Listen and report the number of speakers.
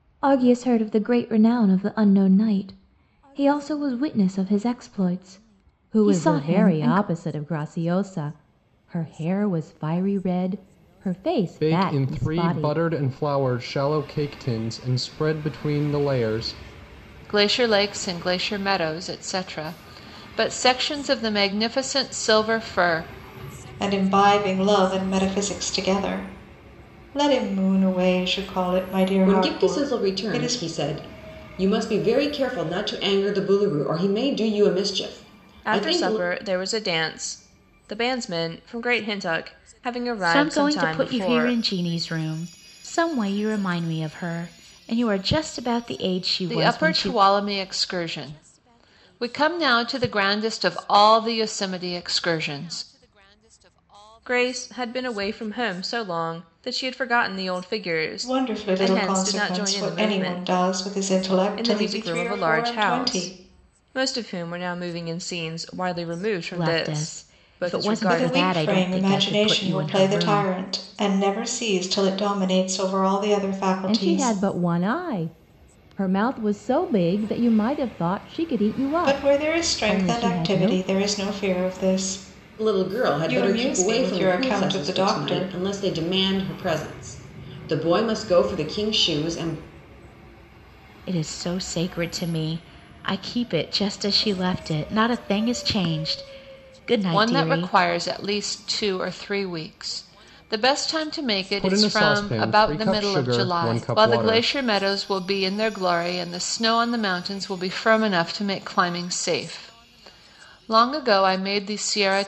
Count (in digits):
8